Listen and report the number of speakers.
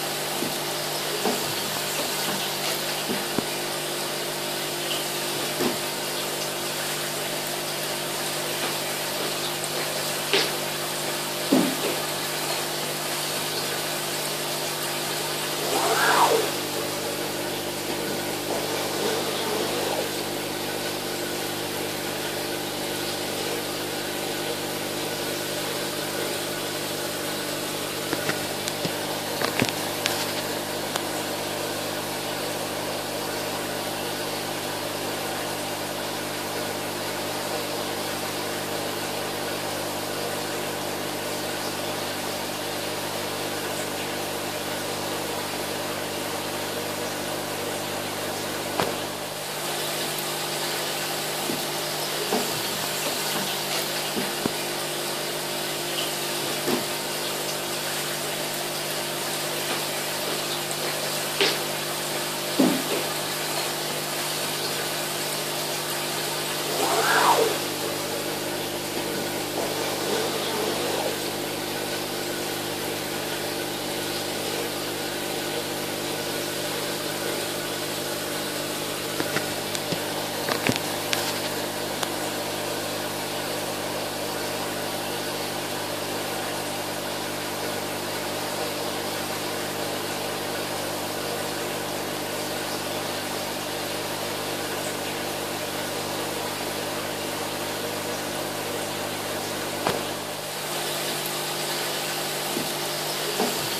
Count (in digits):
0